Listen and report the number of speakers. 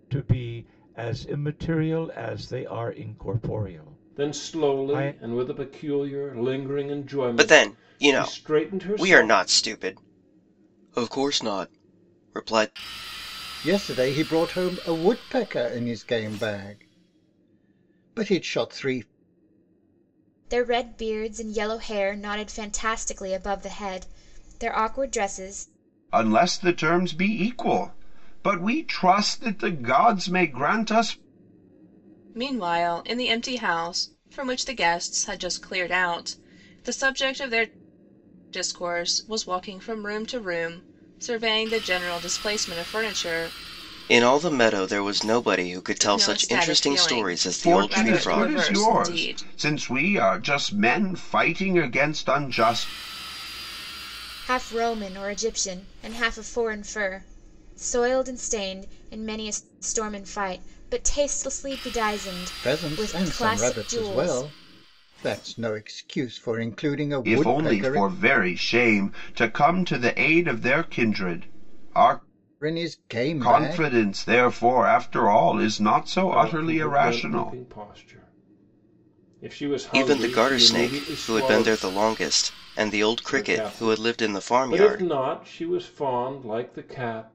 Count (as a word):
seven